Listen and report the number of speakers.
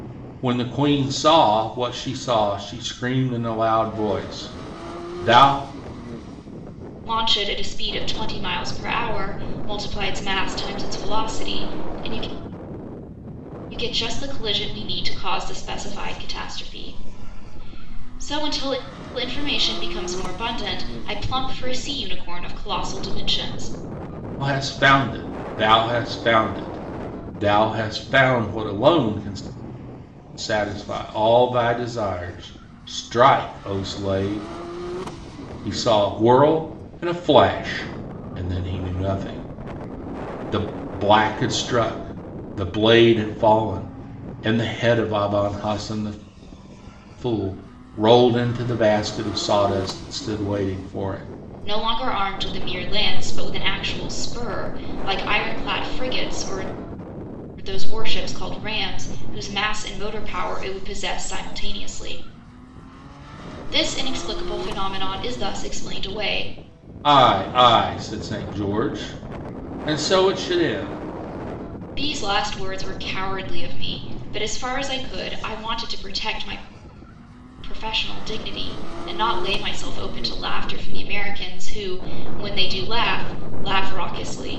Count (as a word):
two